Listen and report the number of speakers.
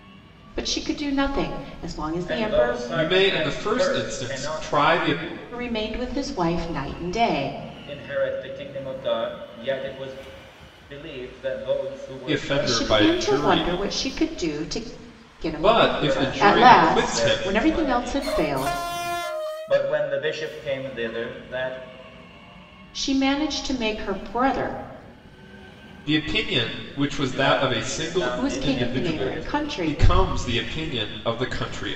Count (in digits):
3